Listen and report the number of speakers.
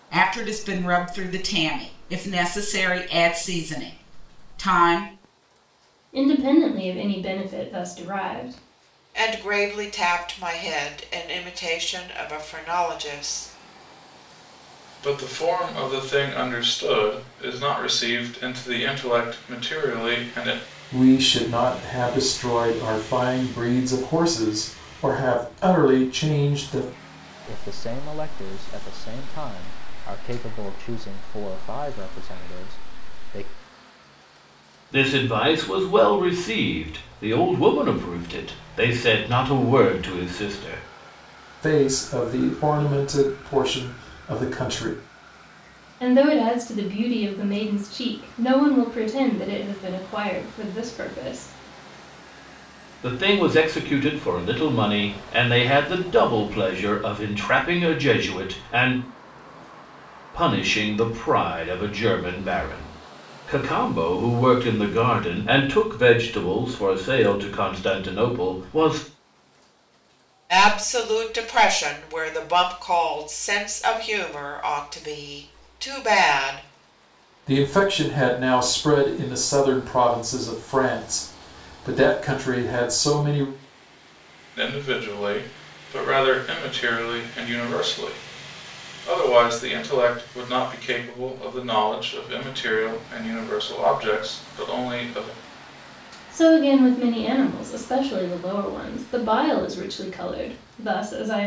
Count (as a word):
seven